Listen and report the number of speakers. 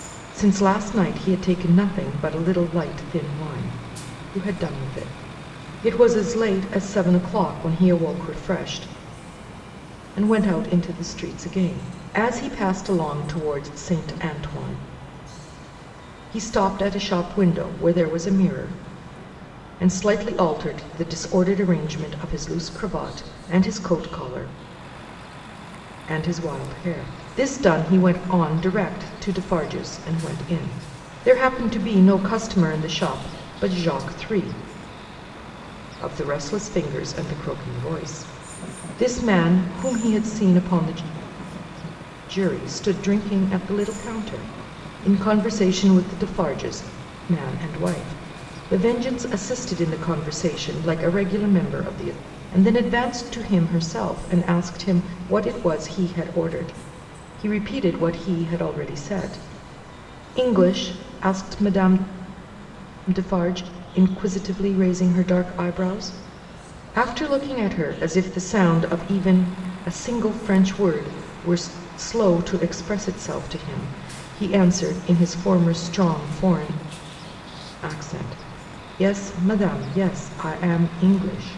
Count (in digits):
1